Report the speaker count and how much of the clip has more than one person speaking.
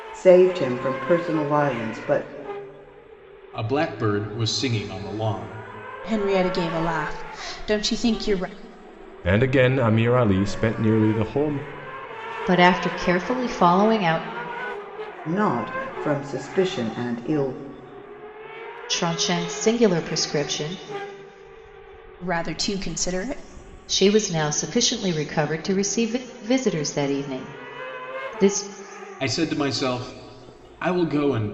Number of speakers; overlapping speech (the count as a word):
five, no overlap